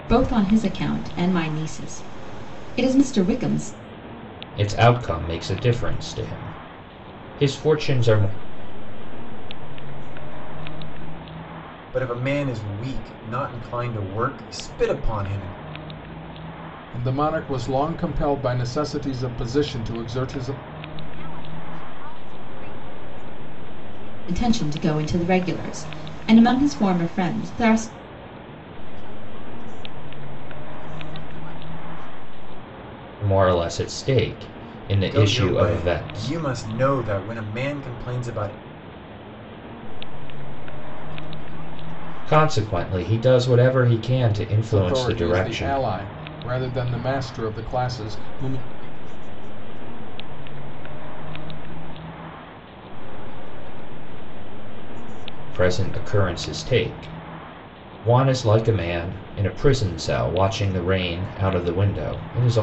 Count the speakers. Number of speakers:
5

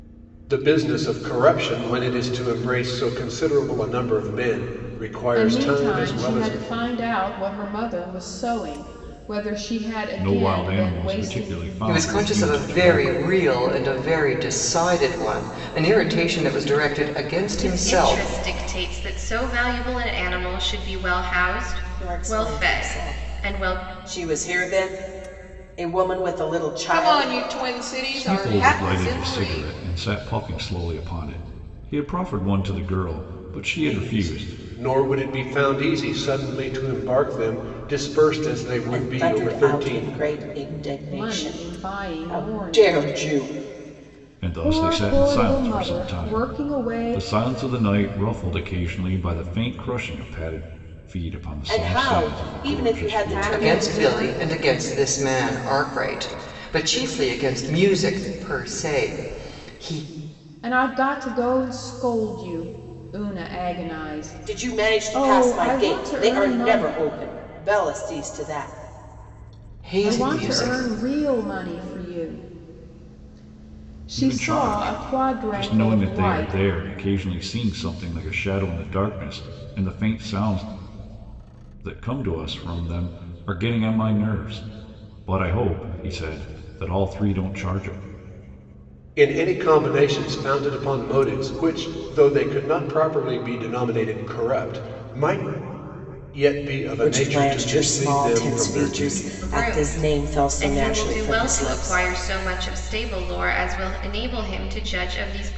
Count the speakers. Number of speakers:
7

